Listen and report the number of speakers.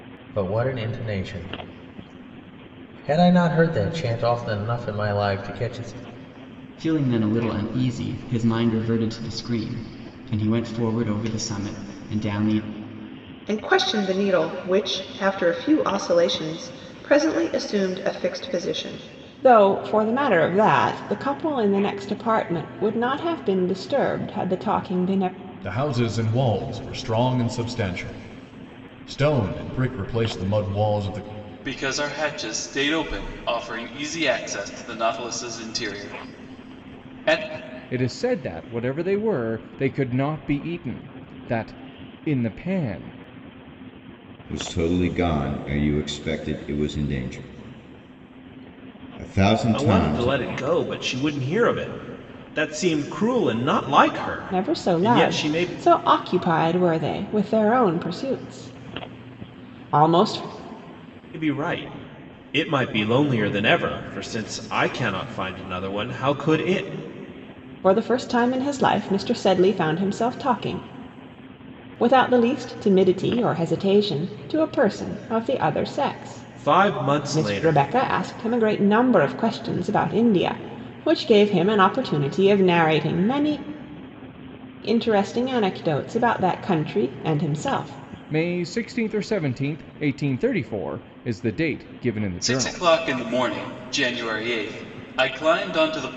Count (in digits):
9